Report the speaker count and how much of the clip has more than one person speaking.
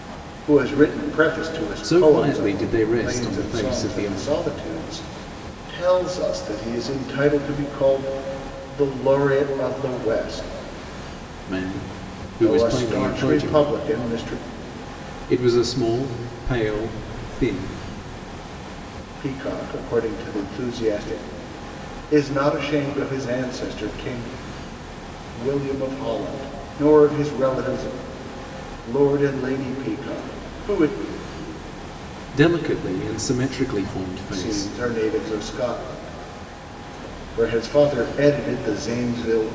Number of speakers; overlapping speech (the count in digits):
2, about 11%